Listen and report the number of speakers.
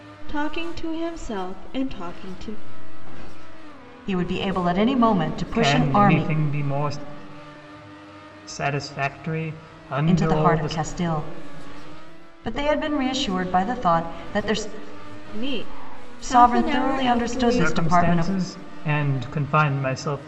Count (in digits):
3